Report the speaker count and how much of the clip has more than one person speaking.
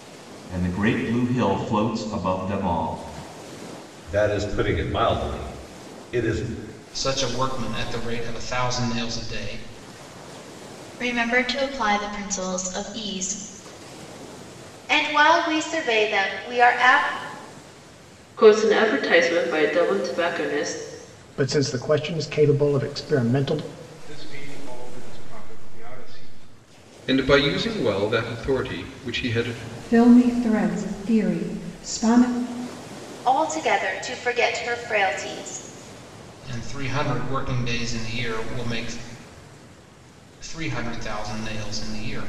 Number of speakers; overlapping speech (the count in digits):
10, no overlap